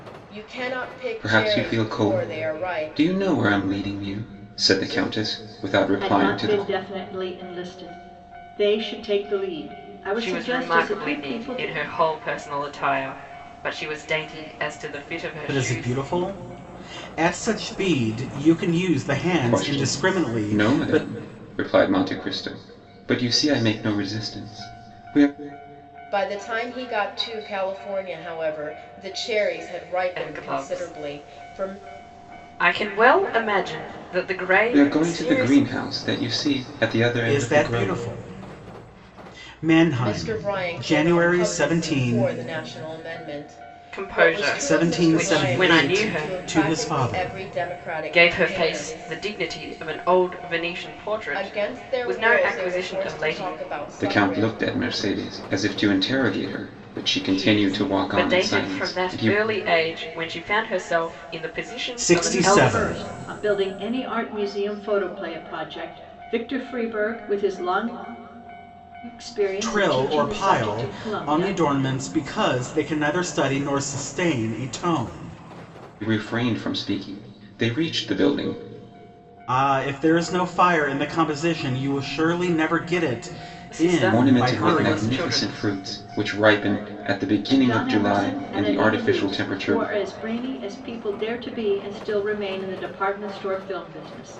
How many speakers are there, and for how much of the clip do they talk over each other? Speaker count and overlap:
5, about 31%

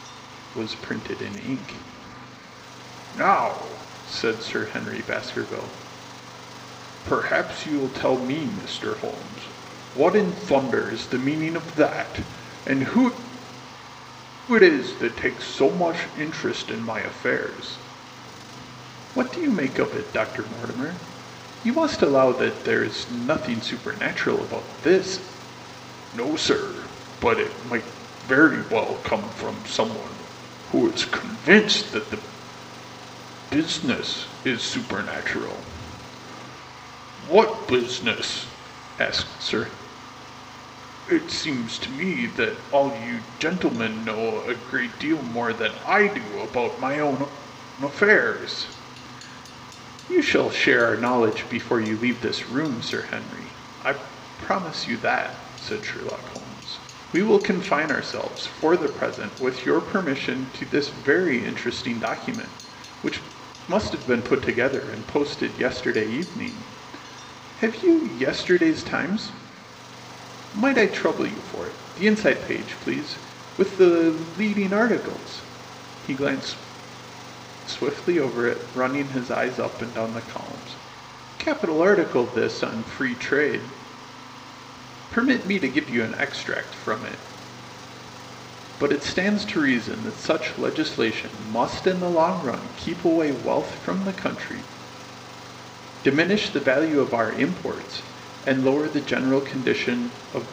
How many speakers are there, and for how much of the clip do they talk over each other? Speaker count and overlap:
1, no overlap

